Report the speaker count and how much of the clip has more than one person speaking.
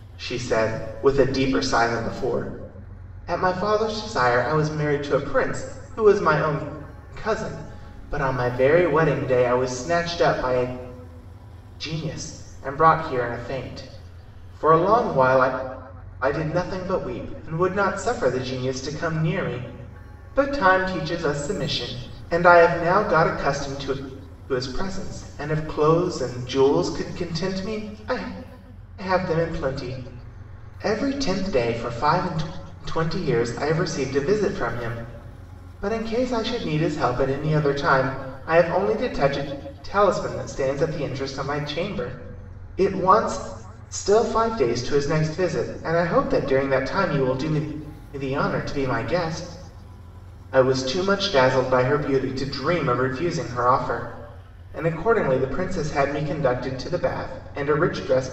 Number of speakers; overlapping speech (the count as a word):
one, no overlap